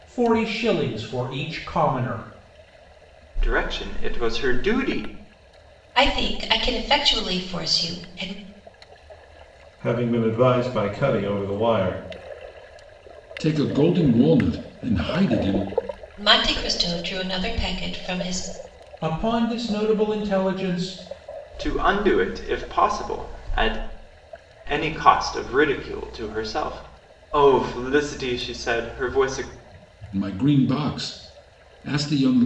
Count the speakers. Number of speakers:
five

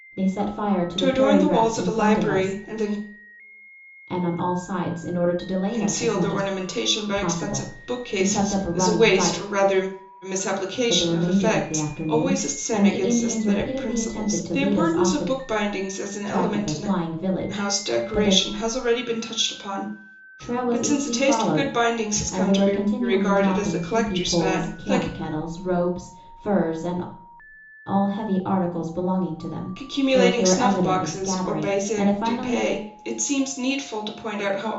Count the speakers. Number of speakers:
two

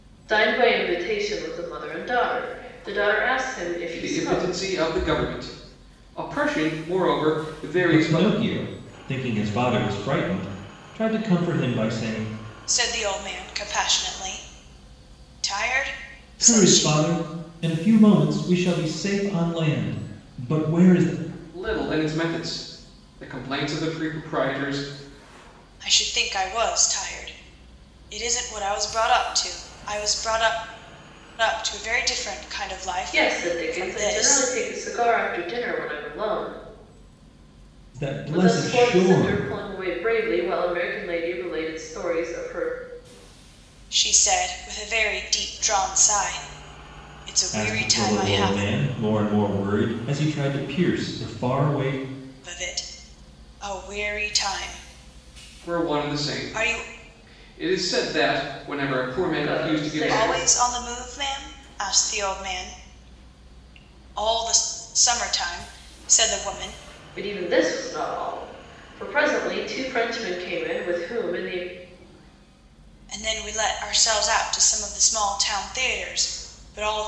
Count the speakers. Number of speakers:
four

